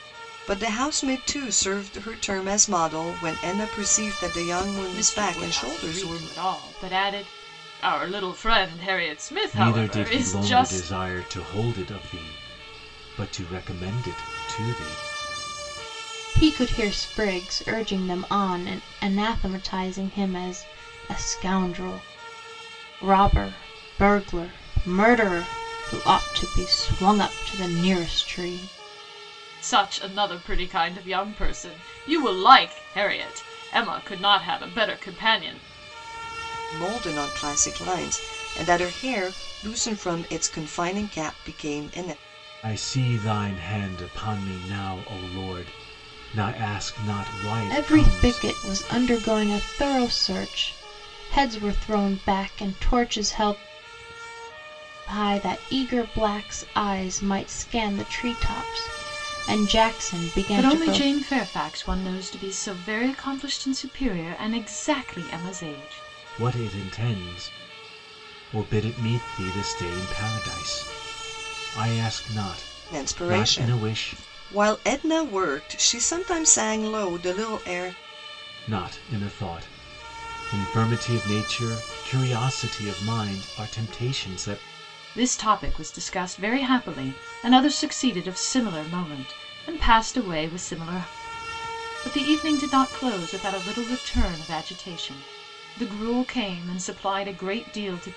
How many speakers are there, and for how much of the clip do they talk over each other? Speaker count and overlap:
4, about 6%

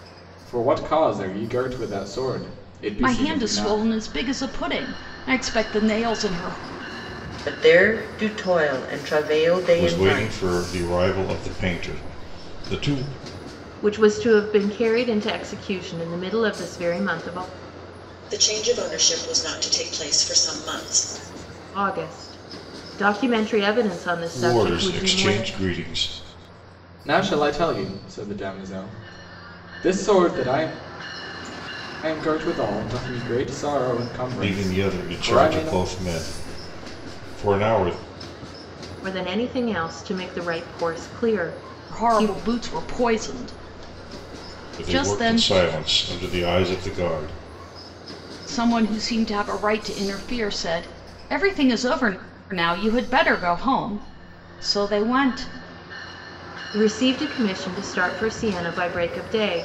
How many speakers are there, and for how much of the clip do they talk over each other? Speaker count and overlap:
6, about 9%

